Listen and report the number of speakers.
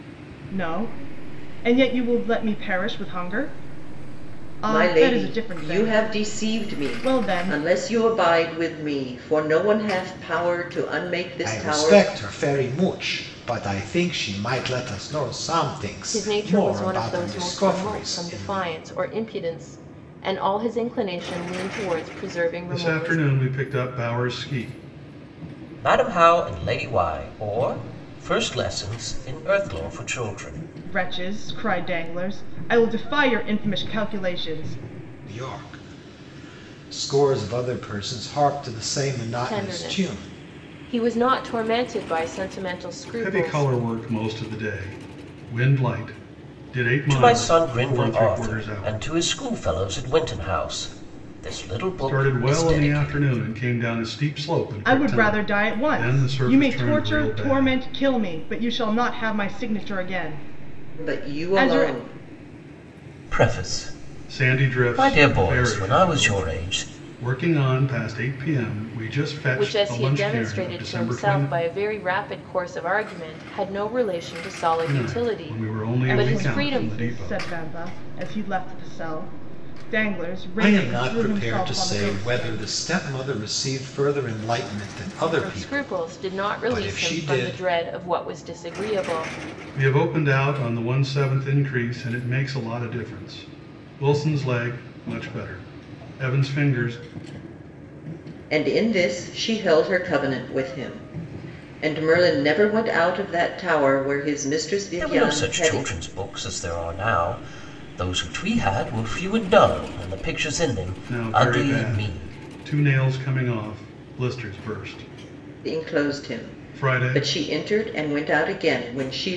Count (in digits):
6